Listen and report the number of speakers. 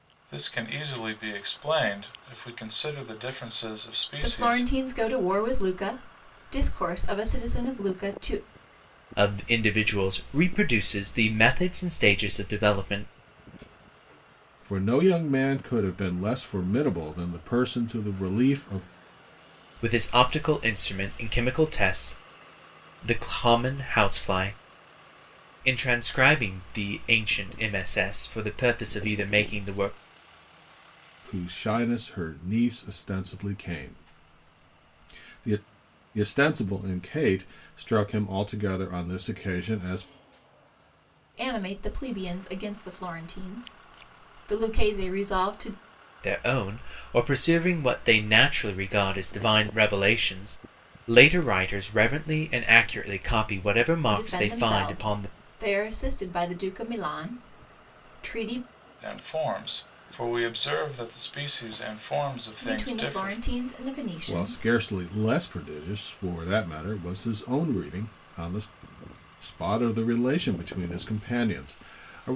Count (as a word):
four